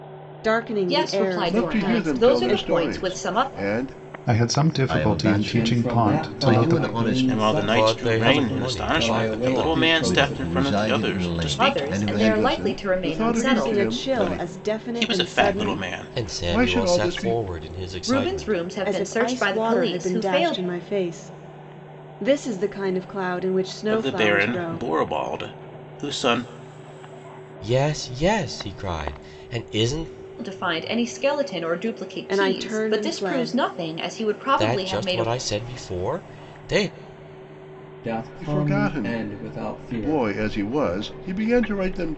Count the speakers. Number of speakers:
8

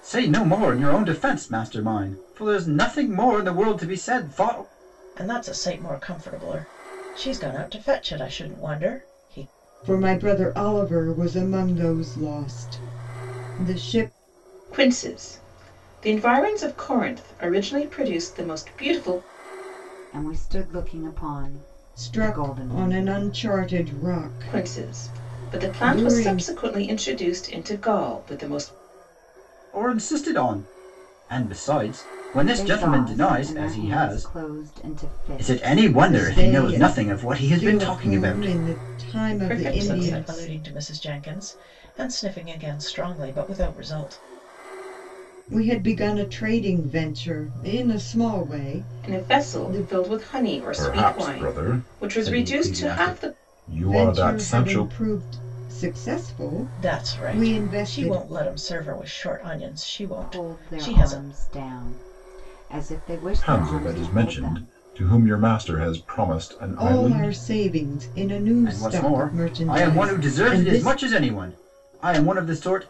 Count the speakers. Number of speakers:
5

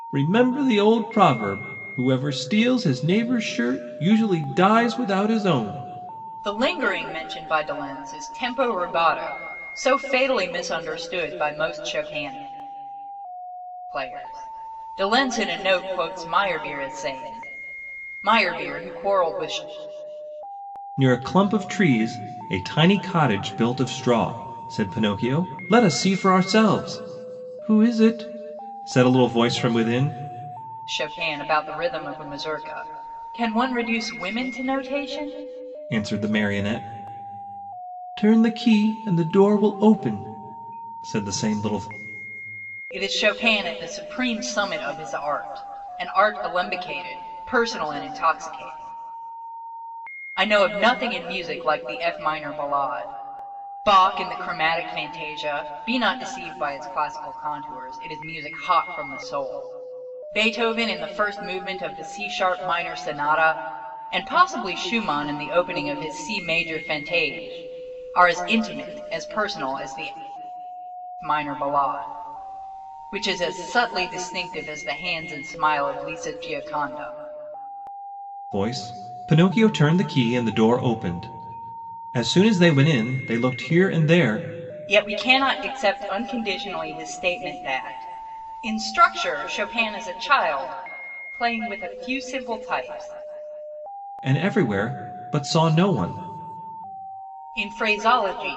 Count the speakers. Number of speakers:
2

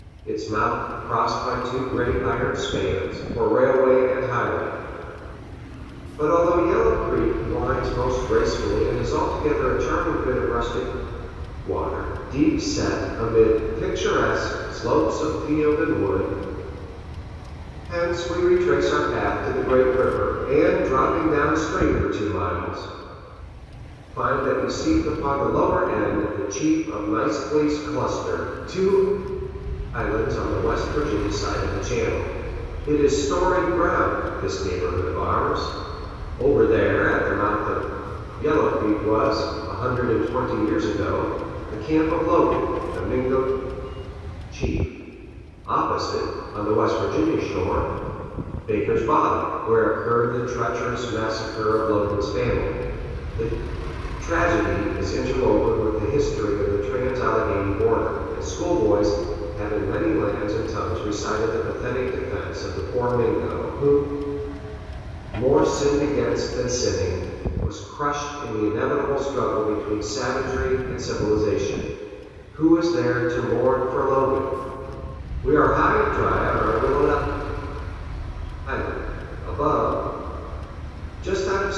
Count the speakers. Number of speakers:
1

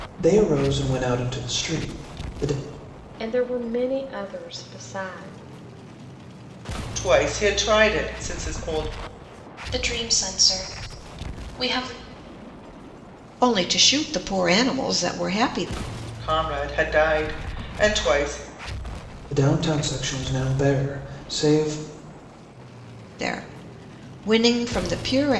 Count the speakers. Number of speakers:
5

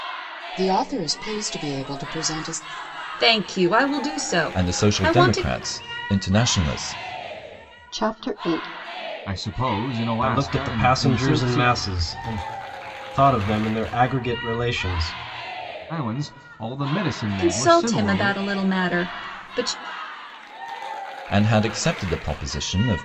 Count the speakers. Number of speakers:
6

